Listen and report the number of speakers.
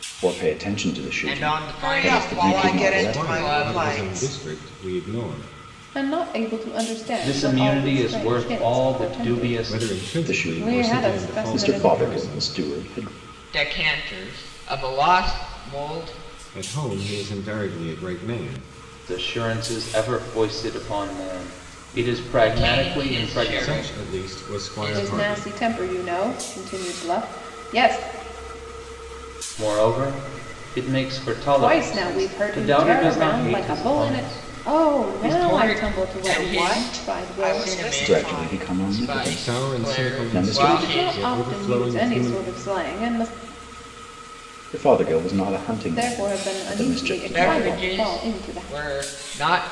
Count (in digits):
6